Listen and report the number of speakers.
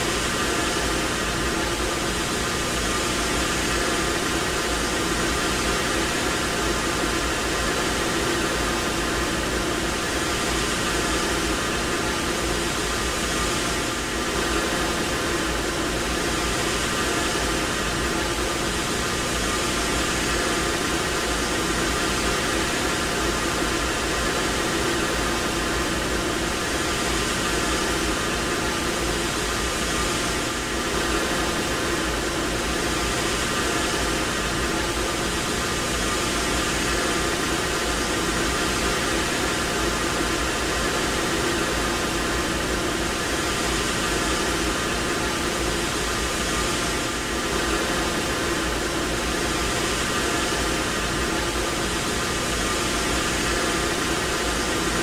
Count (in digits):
0